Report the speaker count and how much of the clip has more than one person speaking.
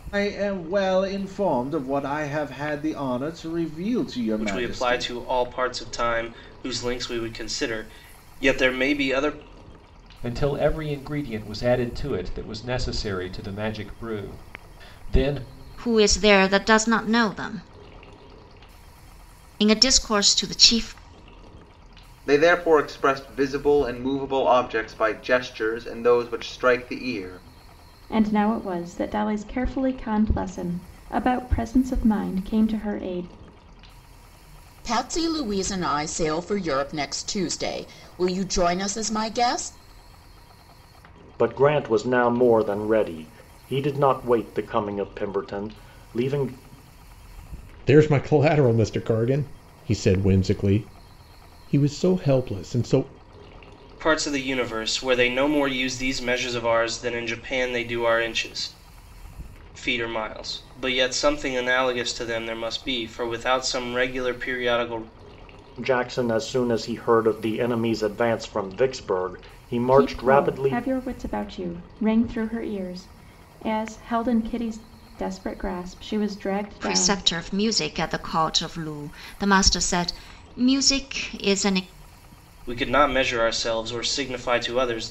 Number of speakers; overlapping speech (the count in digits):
9, about 3%